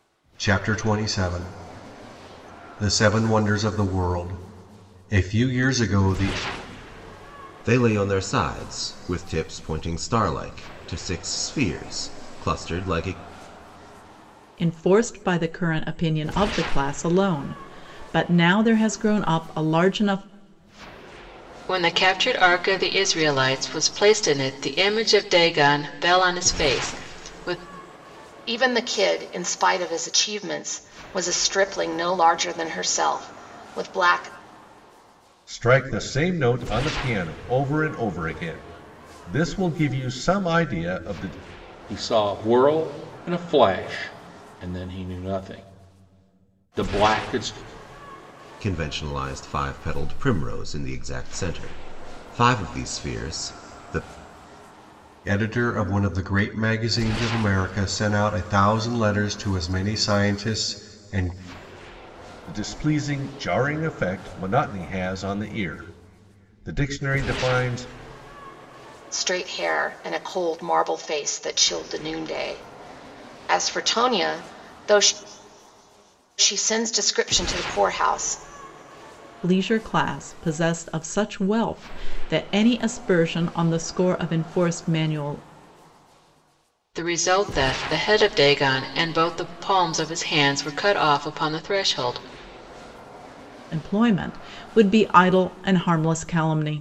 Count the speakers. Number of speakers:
seven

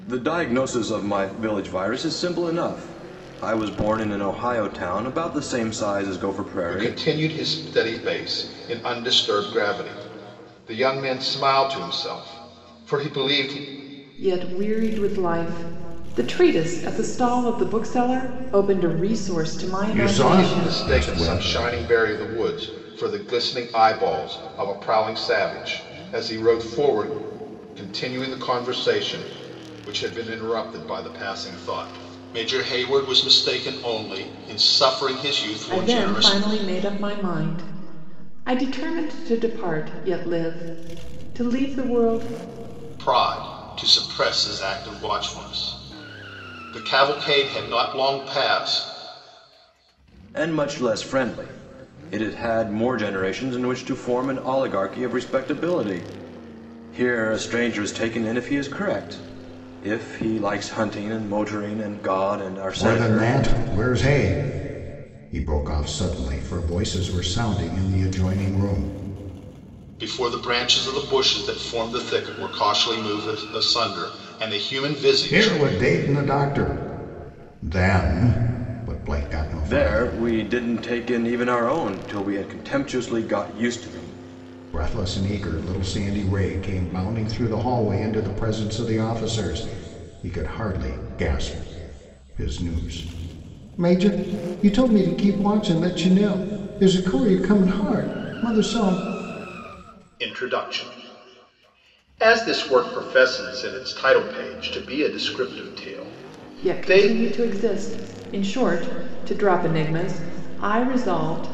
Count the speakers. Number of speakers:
four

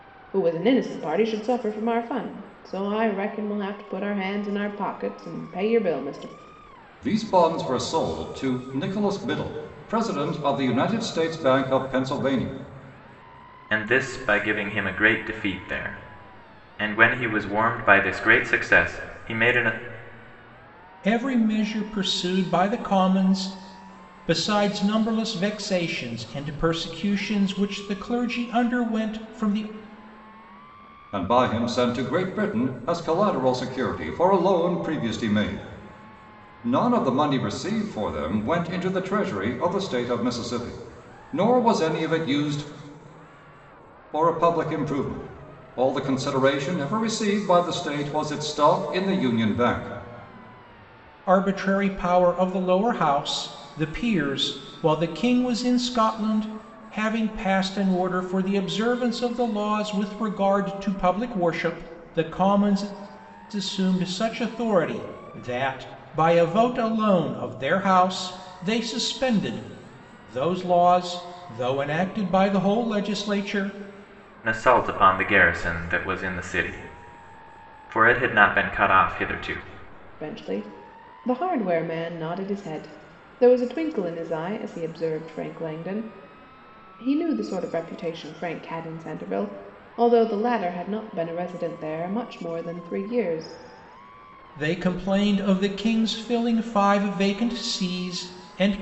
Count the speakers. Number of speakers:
four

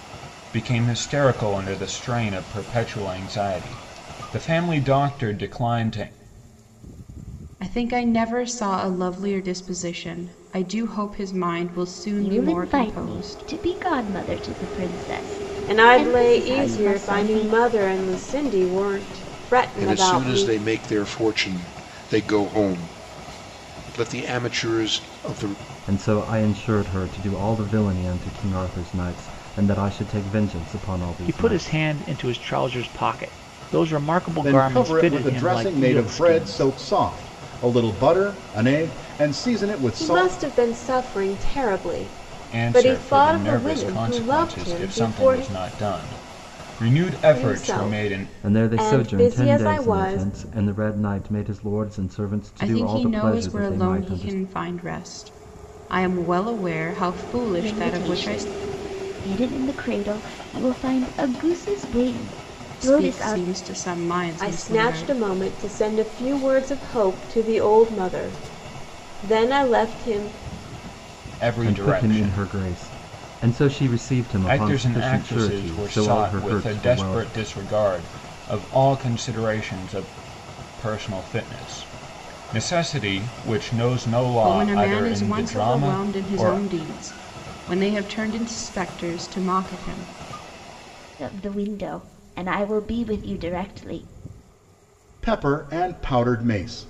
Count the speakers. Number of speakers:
eight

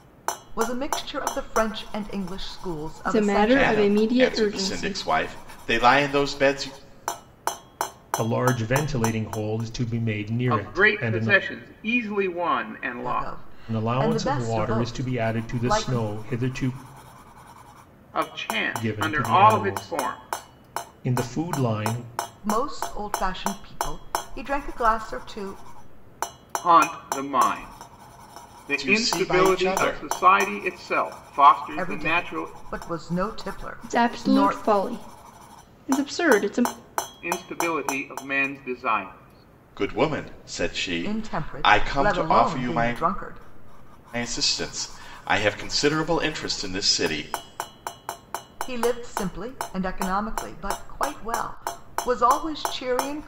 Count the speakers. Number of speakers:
five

